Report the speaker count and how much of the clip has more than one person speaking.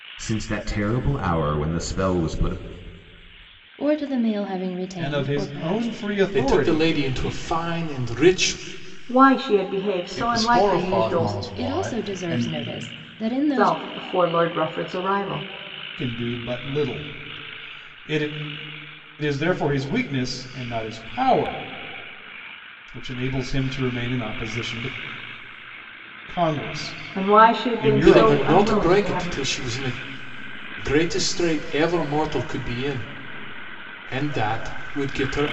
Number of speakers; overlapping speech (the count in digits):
6, about 20%